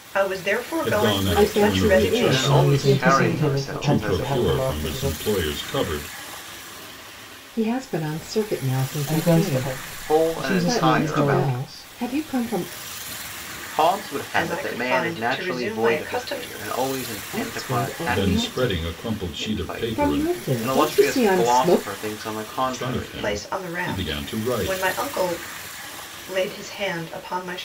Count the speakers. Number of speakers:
five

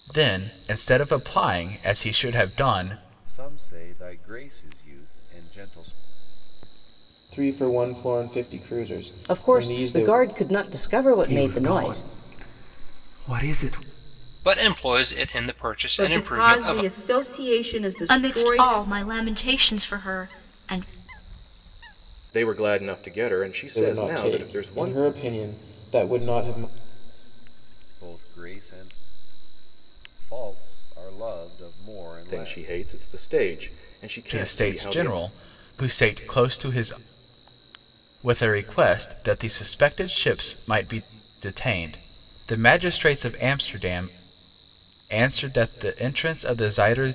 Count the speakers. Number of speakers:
nine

